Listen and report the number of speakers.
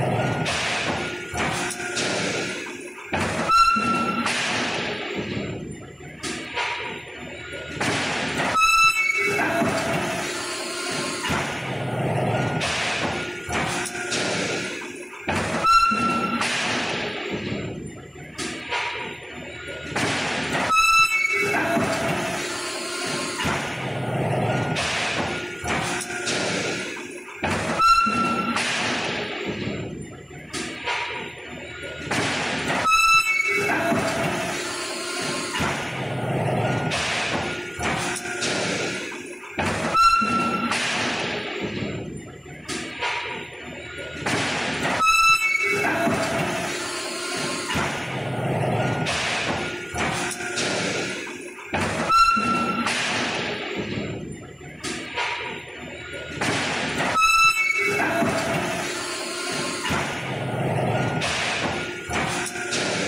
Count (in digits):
0